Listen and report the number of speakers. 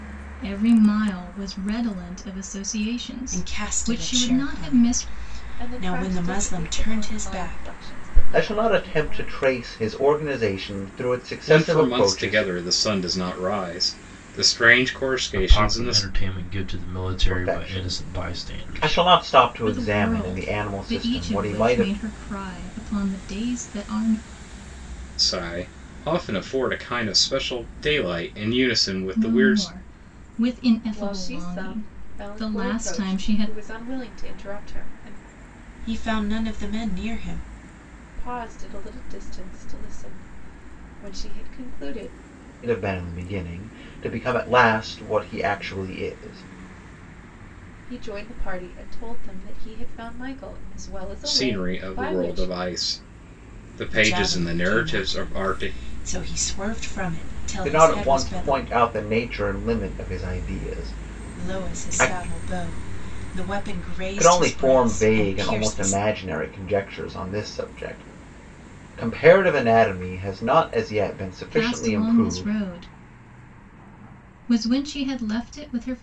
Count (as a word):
six